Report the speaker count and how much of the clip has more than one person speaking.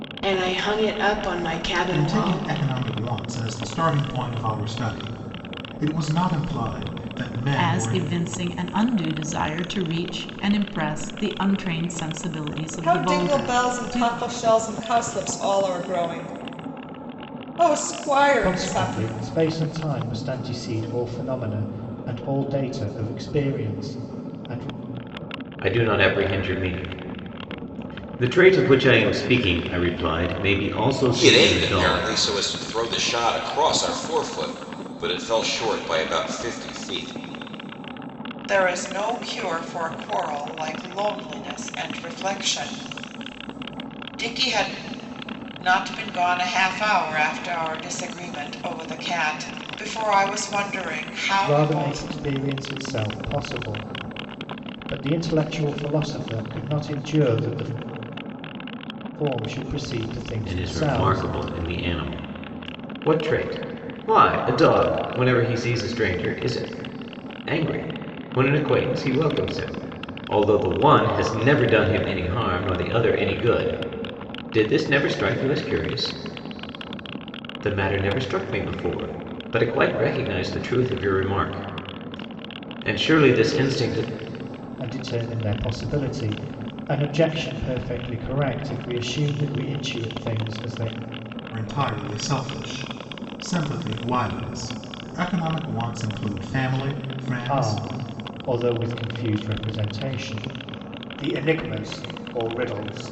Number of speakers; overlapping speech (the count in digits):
8, about 6%